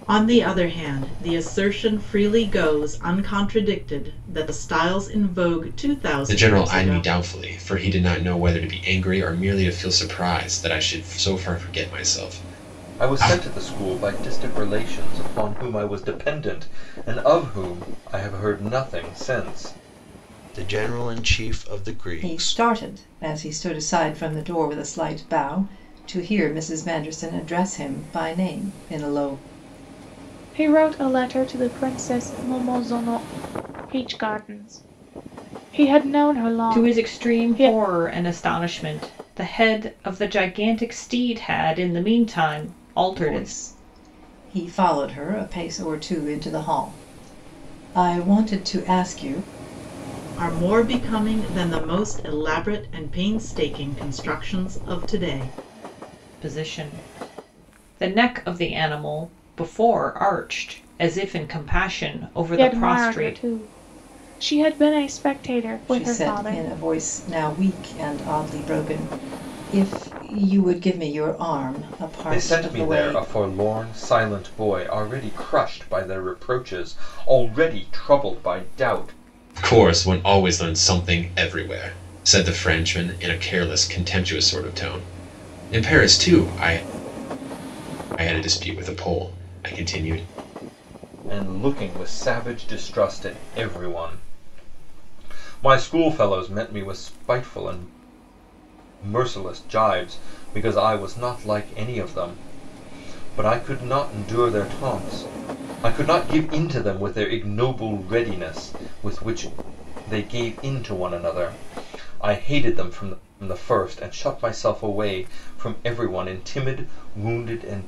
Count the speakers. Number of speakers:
7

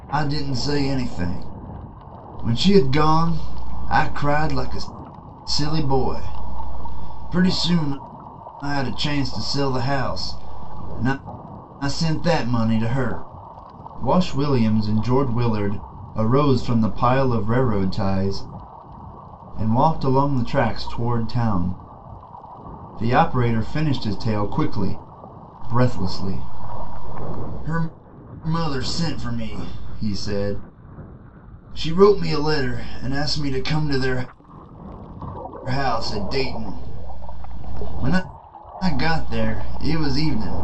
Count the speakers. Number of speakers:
1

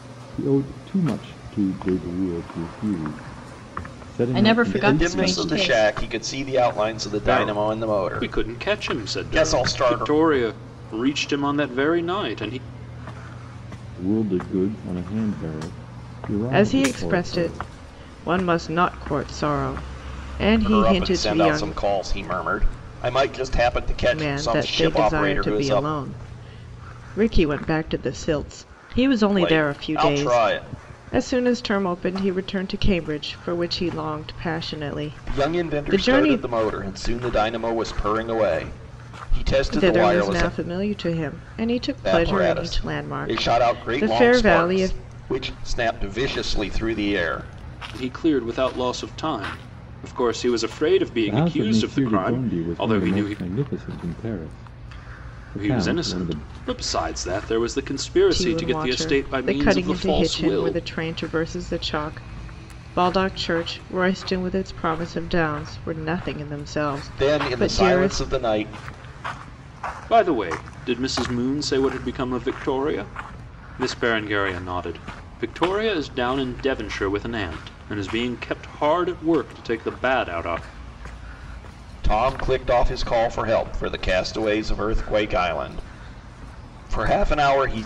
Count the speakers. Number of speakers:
4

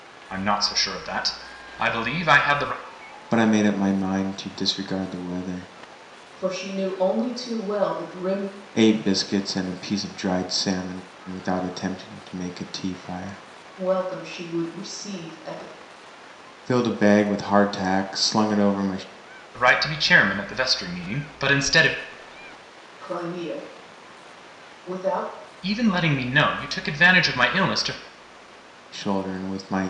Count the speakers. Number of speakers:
3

